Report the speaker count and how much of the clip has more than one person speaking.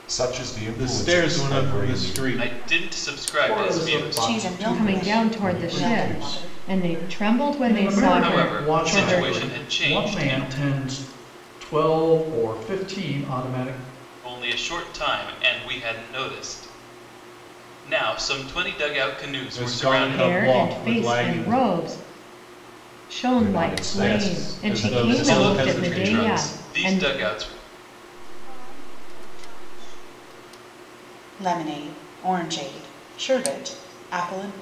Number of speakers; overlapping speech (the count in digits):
7, about 43%